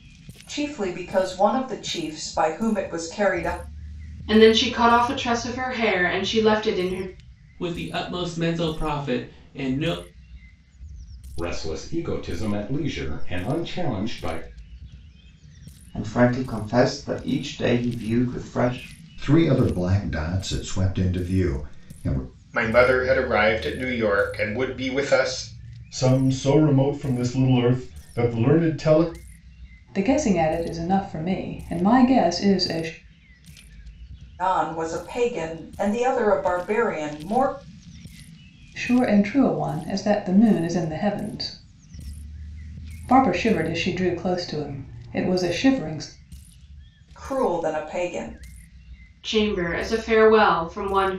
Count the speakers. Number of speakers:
9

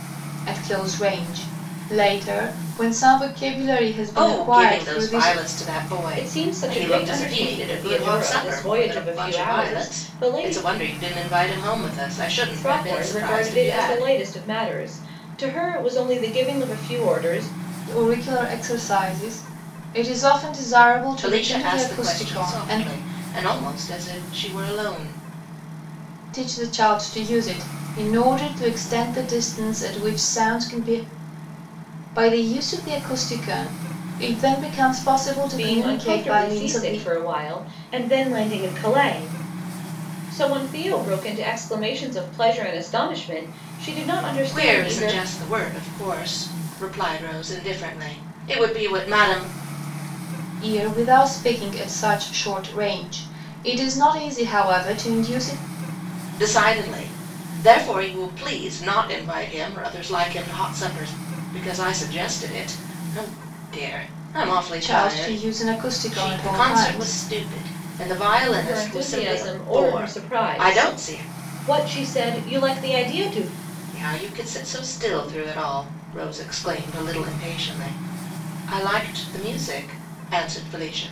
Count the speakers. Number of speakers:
3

